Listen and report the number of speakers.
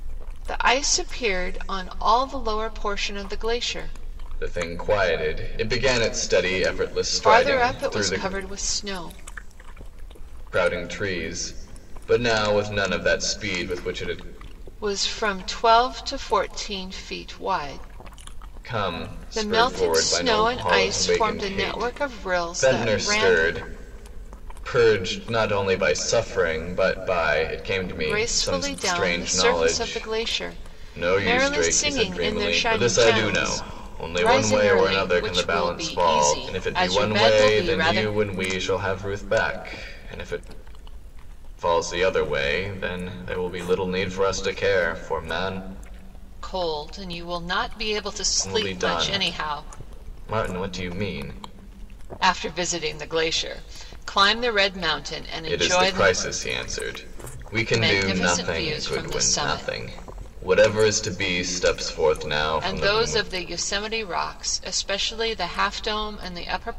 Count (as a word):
two